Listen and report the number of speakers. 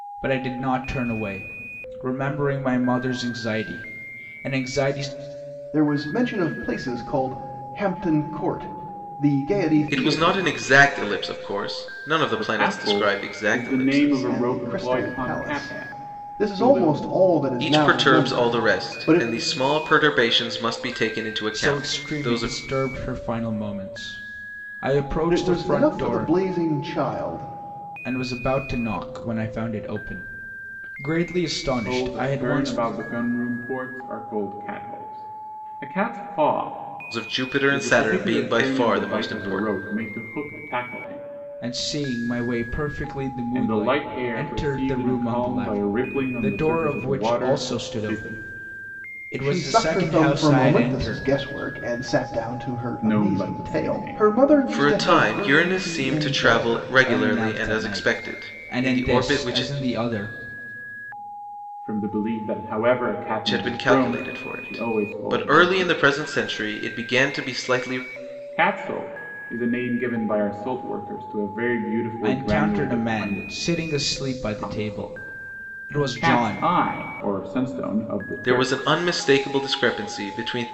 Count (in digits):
4